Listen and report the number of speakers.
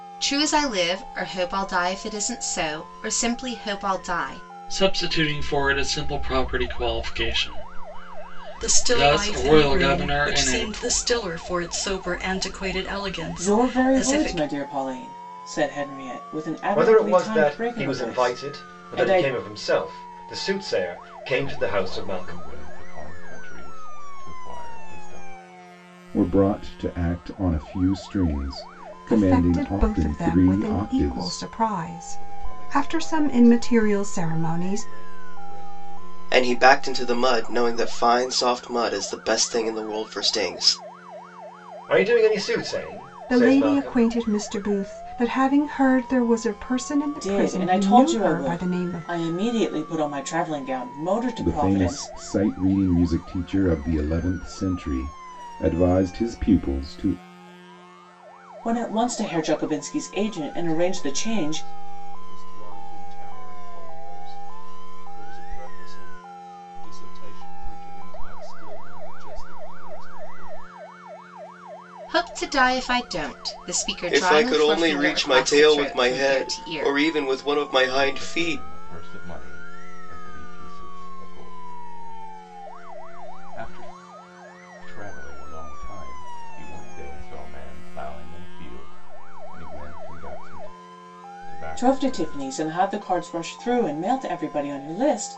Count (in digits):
10